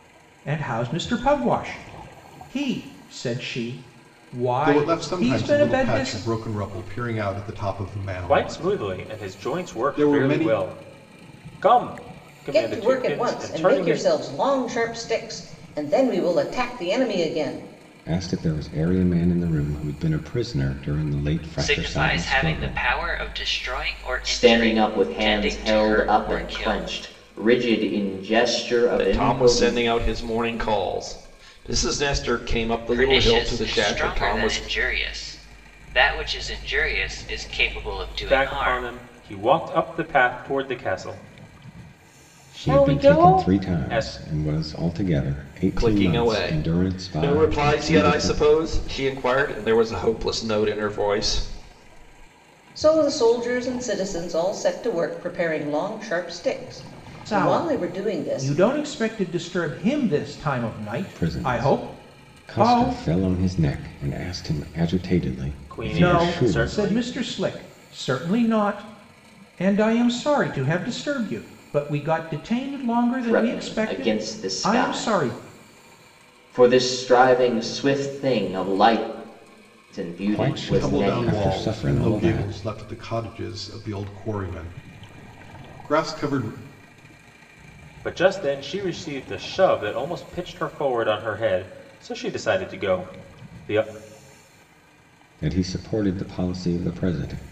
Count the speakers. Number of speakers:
8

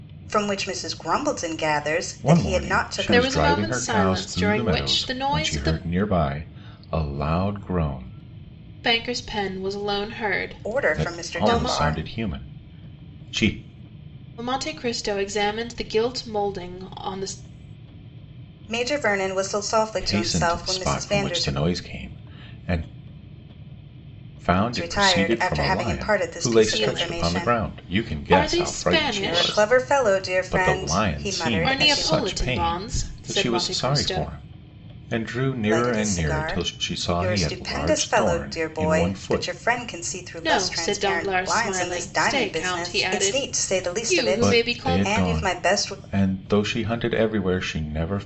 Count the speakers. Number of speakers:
3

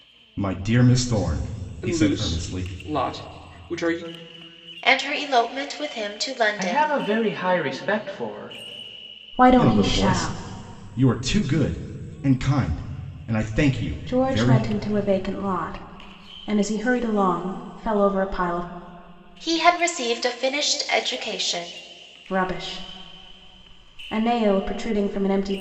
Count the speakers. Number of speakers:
5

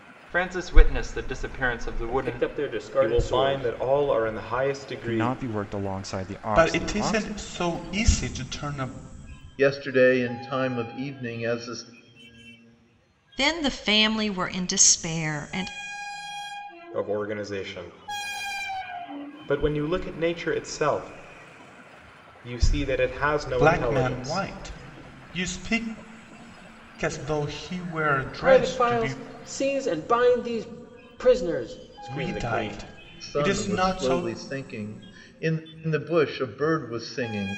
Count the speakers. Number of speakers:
7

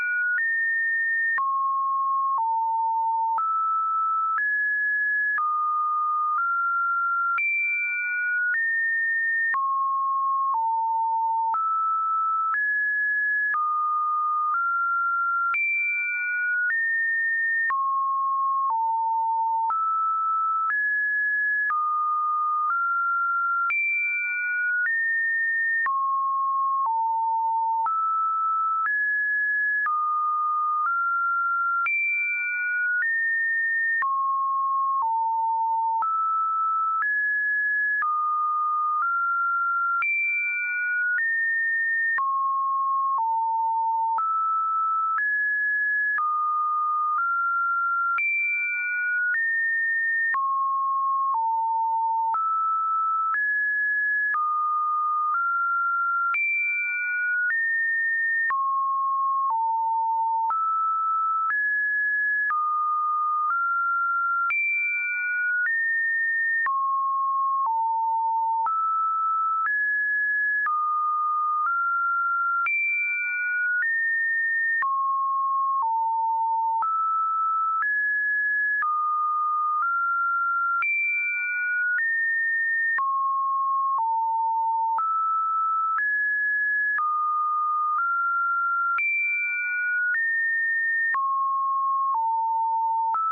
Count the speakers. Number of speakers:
0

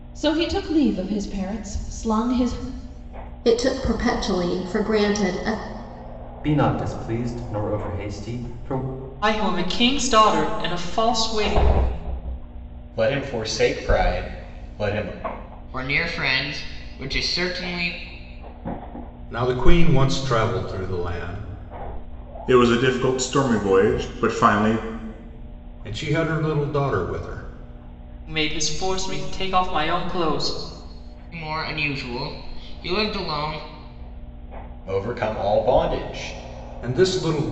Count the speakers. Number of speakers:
8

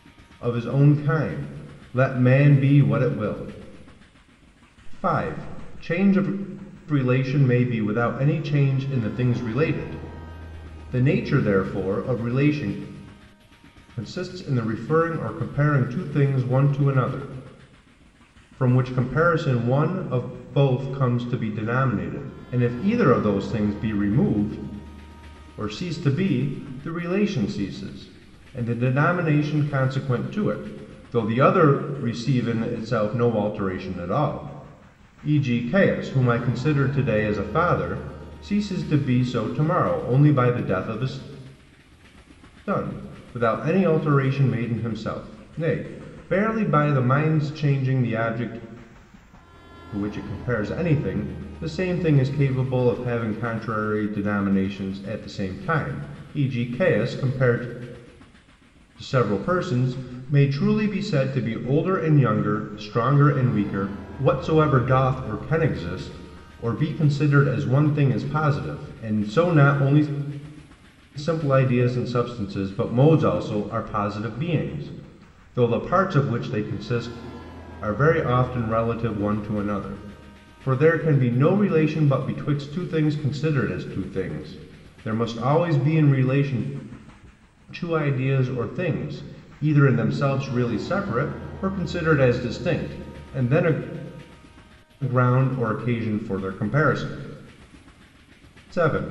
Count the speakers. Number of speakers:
1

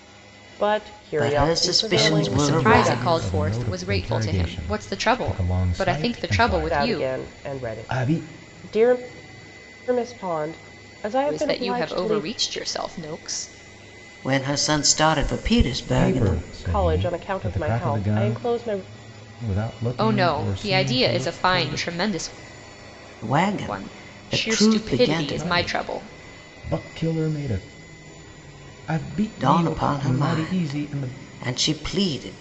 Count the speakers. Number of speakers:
4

